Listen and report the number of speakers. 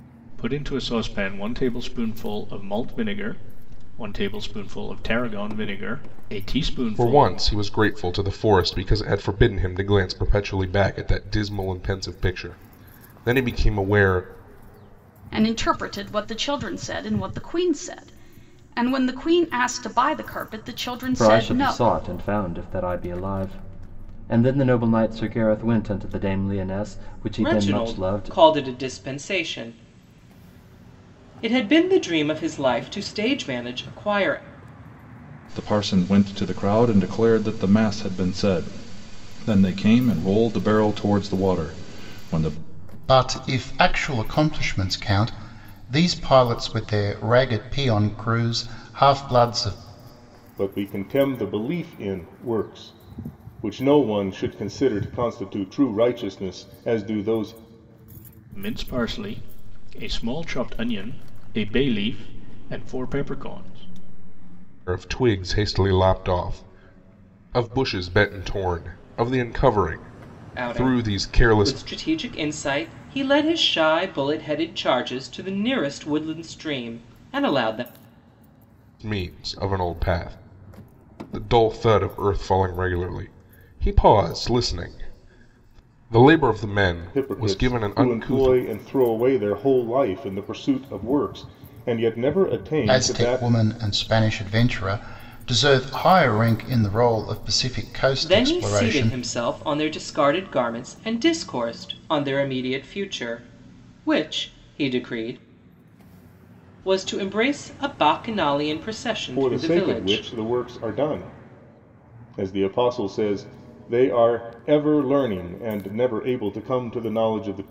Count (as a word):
eight